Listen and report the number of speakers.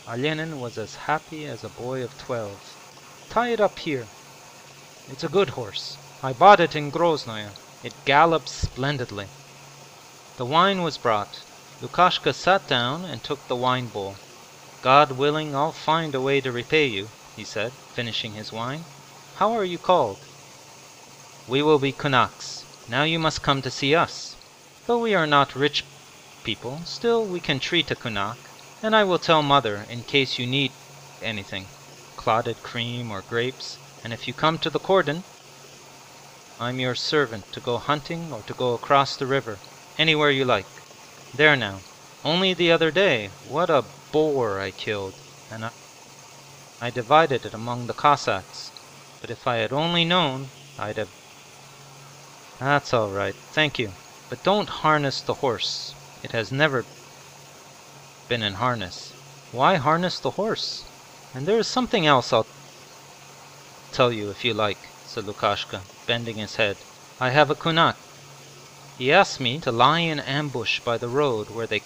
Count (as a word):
one